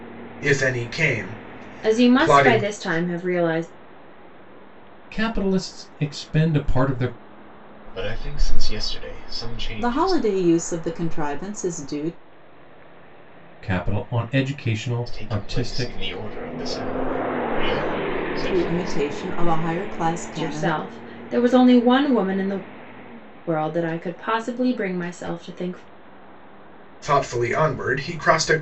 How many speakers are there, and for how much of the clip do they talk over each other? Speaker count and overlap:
5, about 12%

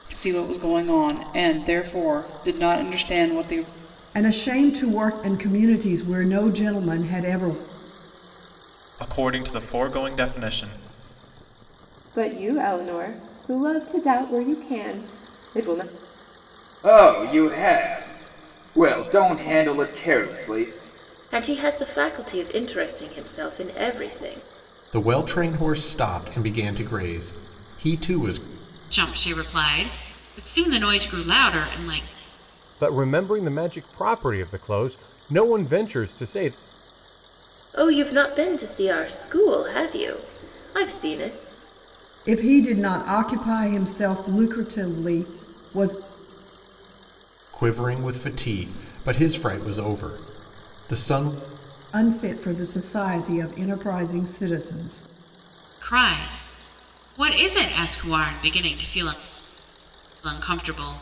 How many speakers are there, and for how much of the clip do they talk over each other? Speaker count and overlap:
9, no overlap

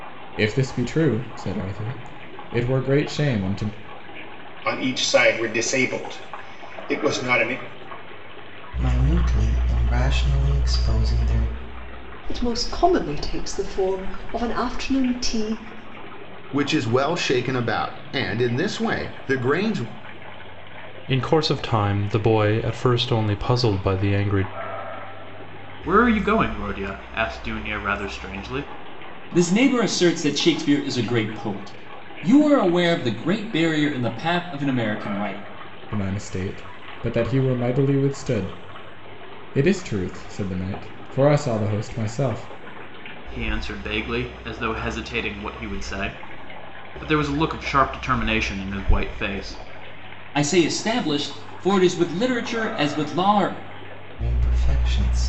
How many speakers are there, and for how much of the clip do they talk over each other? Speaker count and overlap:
8, no overlap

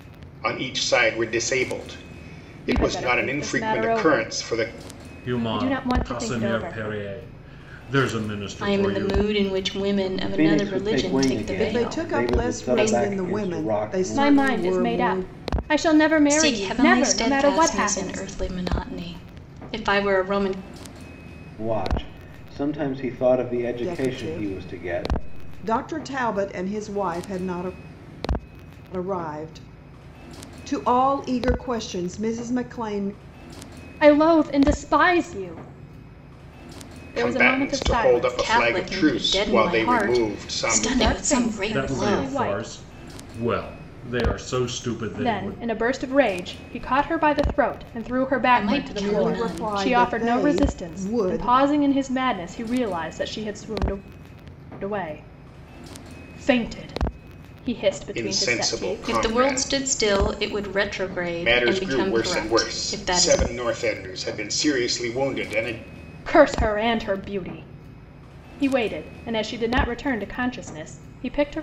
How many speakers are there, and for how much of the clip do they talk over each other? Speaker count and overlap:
6, about 36%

